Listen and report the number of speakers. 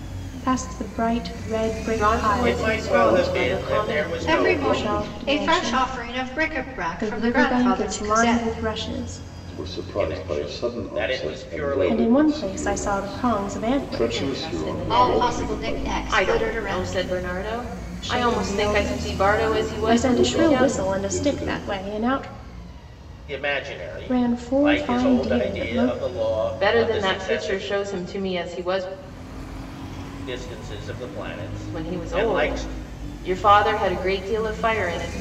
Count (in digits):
5